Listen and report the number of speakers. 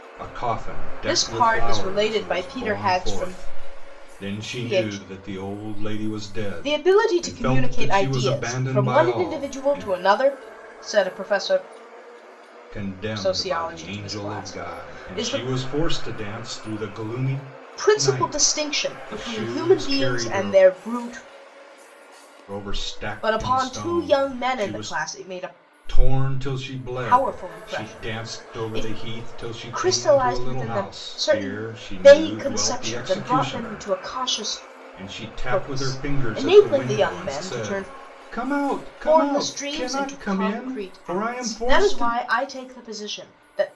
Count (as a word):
two